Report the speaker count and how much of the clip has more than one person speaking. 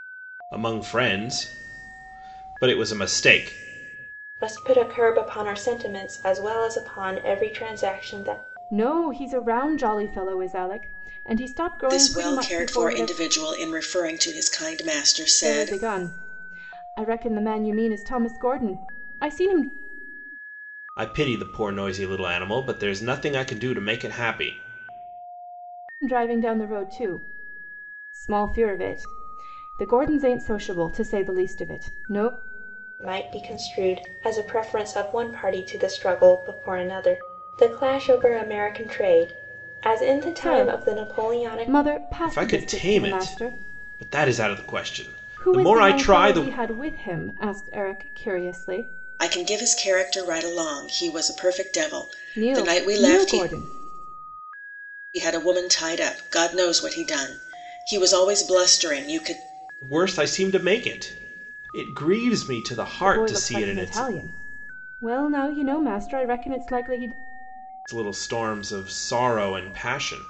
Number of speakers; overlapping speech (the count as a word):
four, about 11%